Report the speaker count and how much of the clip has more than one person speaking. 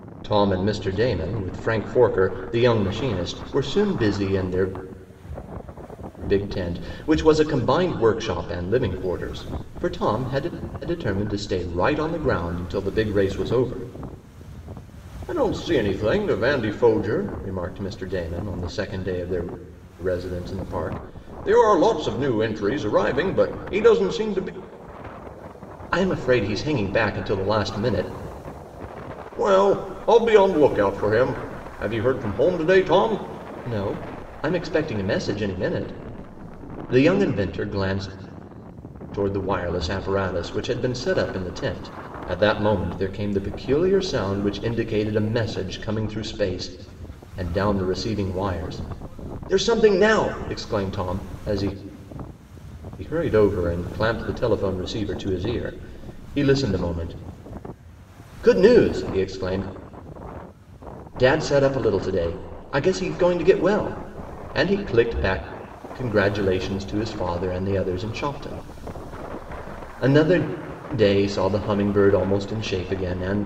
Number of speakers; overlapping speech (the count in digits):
1, no overlap